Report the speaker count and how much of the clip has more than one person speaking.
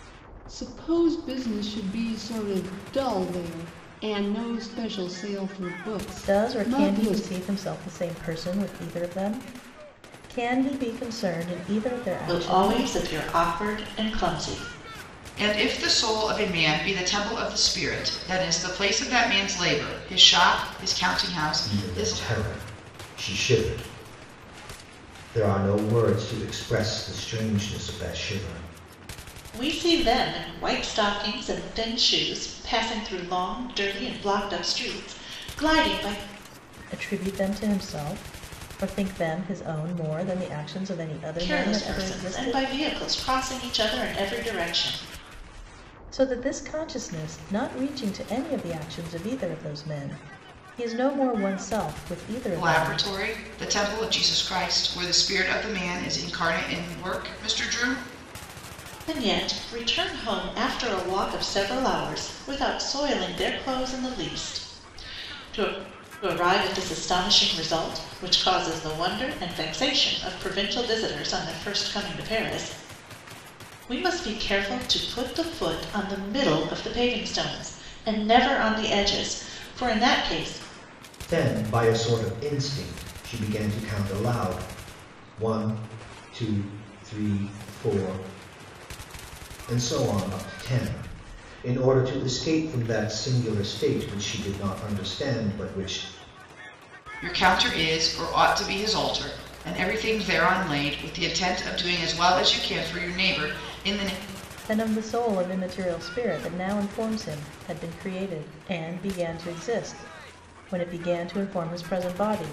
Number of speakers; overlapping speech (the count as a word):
five, about 4%